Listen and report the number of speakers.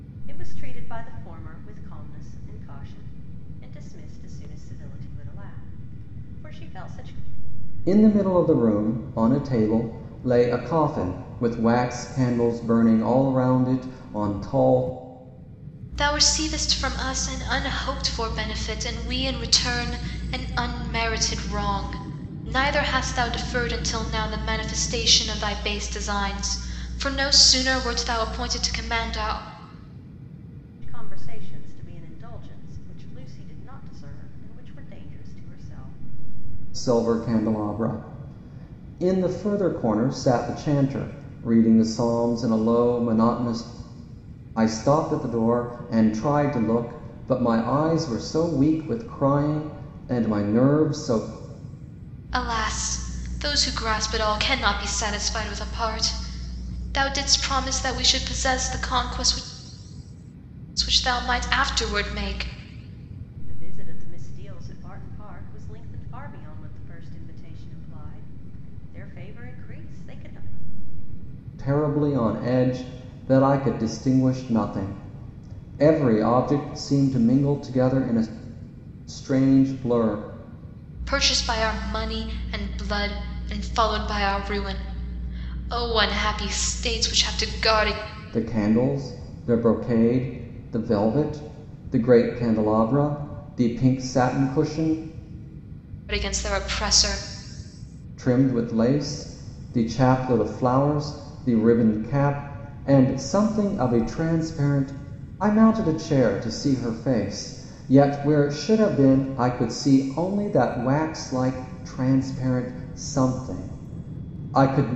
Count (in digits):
3